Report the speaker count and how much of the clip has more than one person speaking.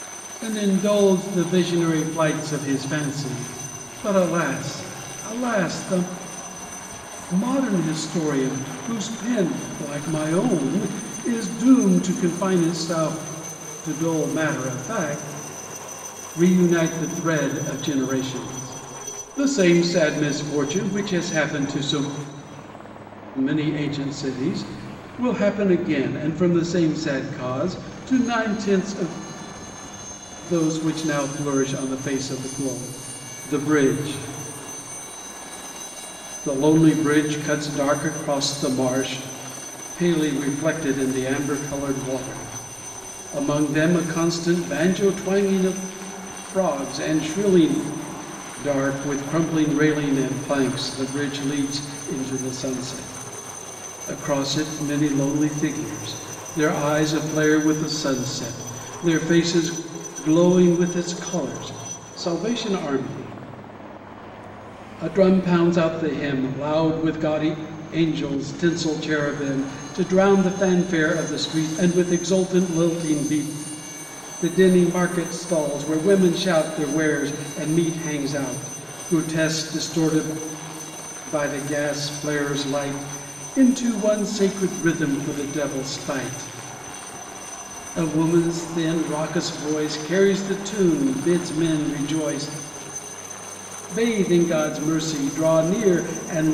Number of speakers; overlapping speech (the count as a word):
one, no overlap